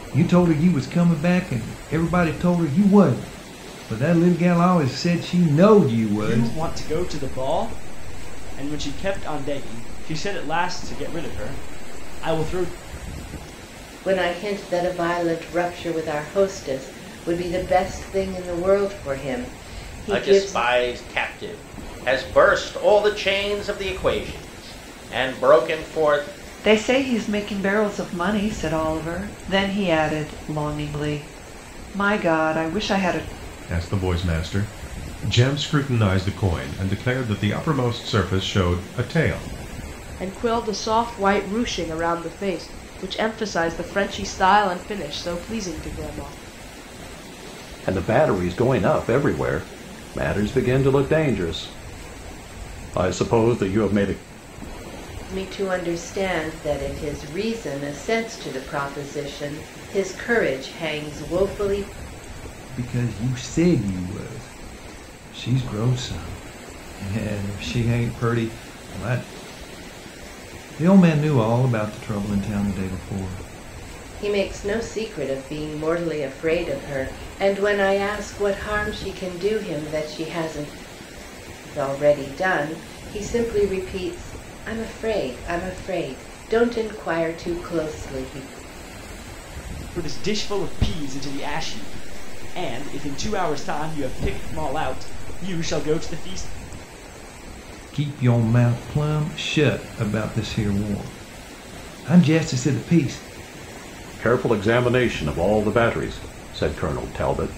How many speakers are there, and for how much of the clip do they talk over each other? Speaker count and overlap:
eight, about 1%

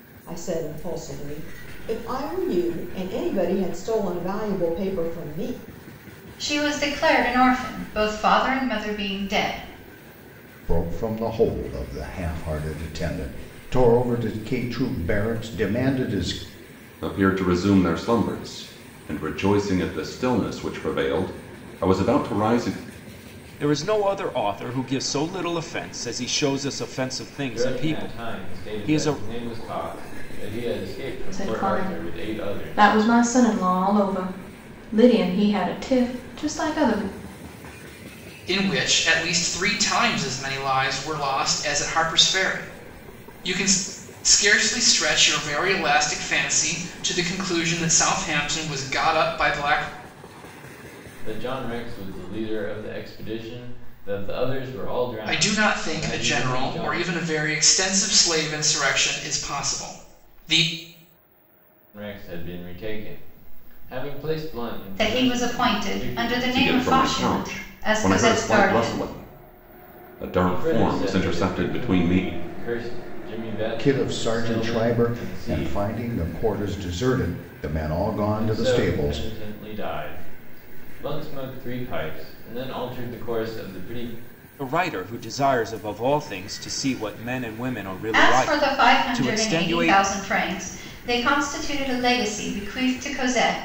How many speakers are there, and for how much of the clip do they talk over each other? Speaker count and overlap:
eight, about 17%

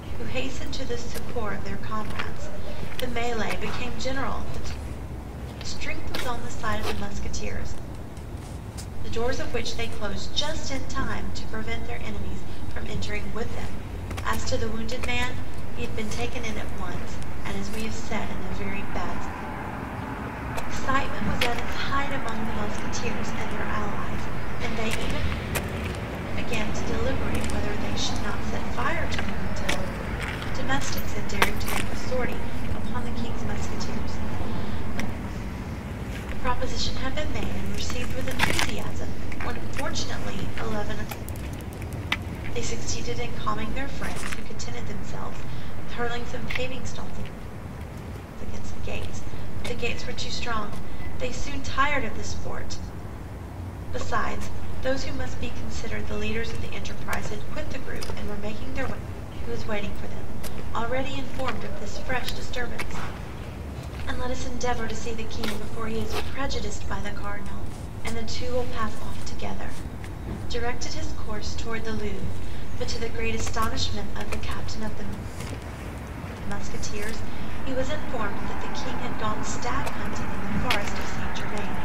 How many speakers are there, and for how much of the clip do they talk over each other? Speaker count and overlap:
one, no overlap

